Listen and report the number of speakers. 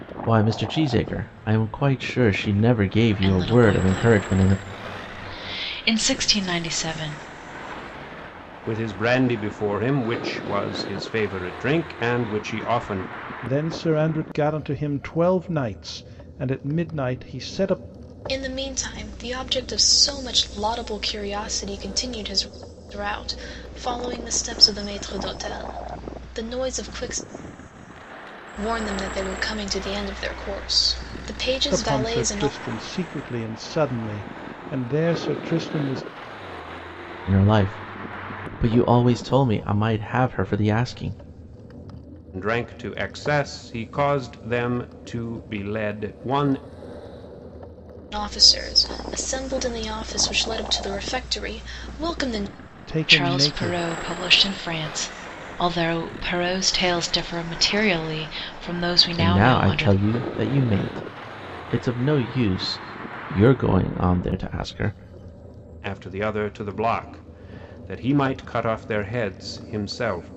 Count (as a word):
five